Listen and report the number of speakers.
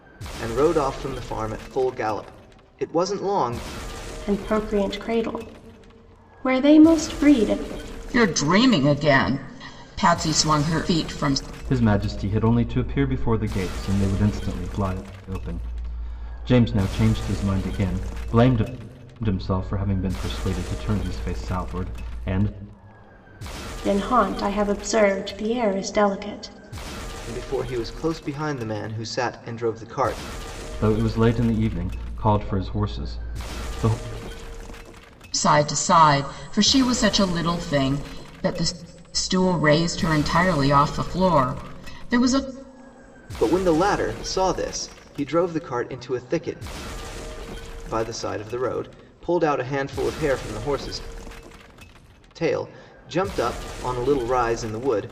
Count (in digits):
4